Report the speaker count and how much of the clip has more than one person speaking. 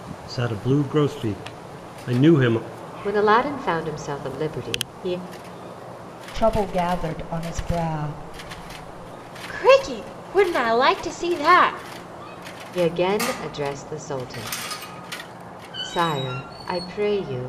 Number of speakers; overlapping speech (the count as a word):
four, no overlap